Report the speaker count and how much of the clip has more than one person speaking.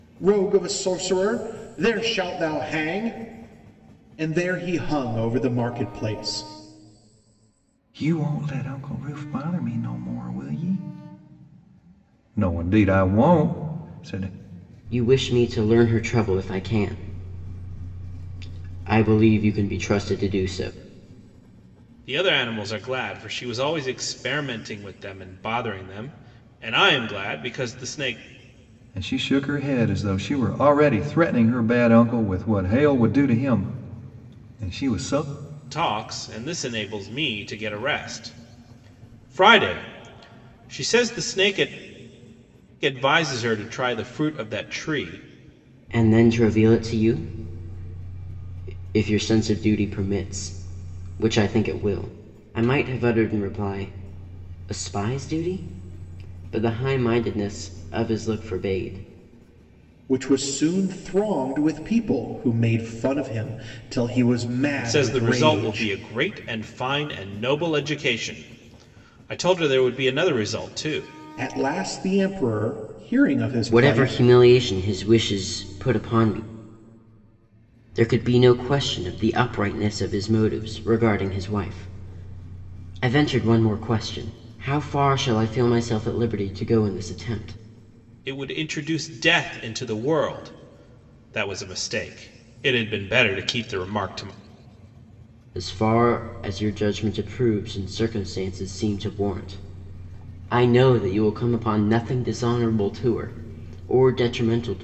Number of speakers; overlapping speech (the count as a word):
four, about 2%